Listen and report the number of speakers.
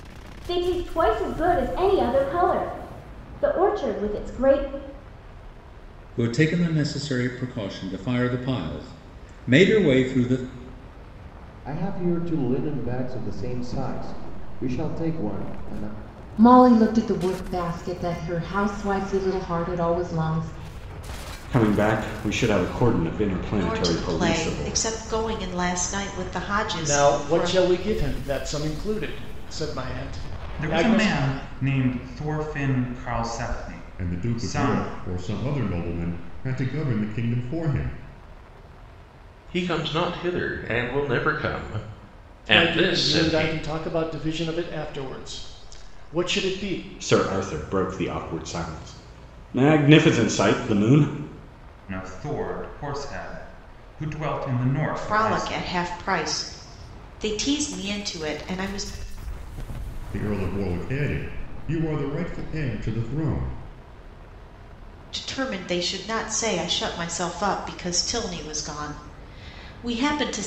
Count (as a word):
ten